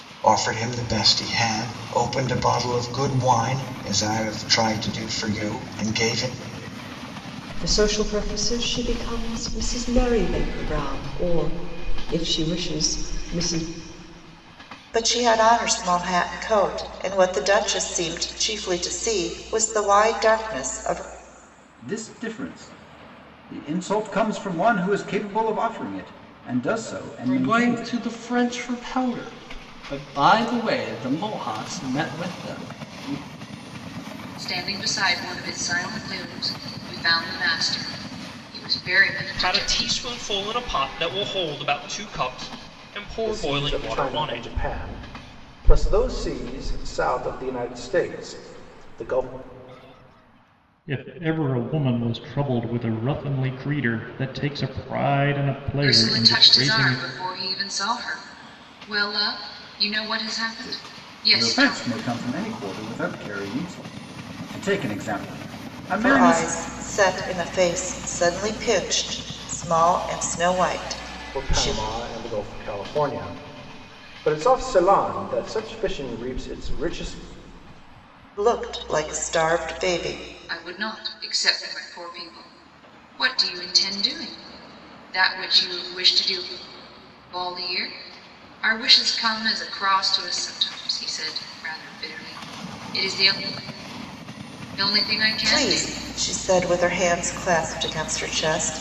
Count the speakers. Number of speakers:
9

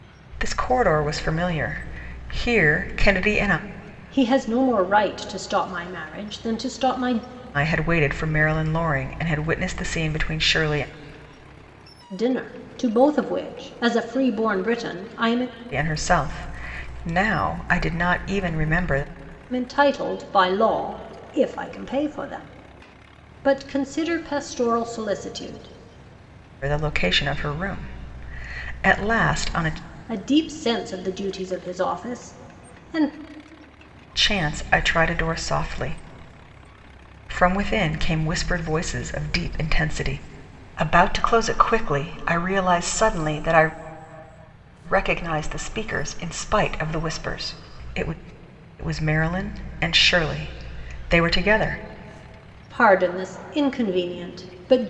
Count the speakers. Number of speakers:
2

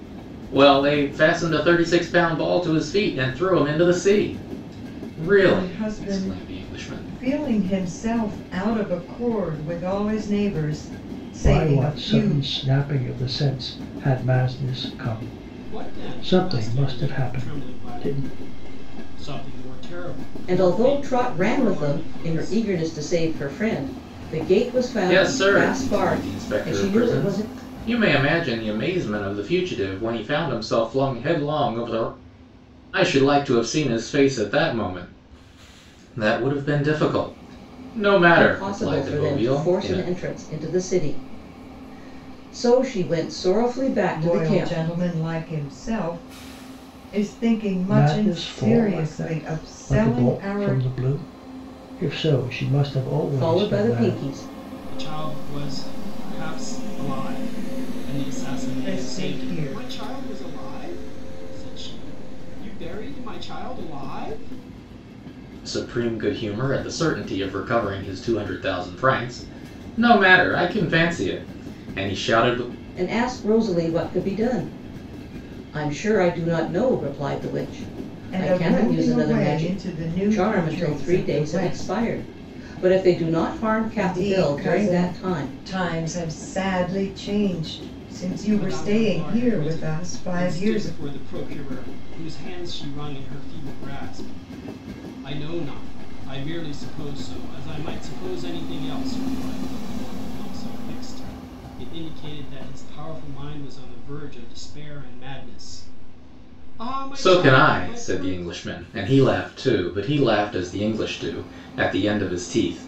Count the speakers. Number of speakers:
5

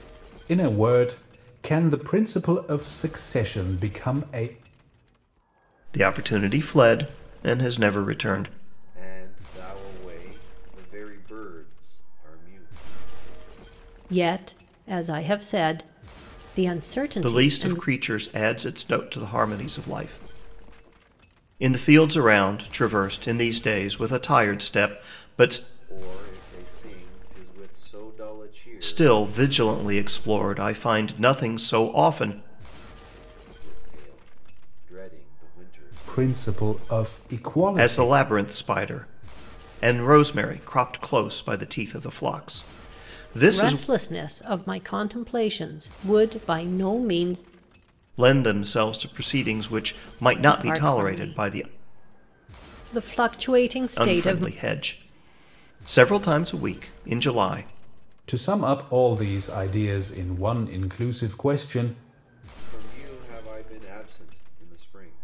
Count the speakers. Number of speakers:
4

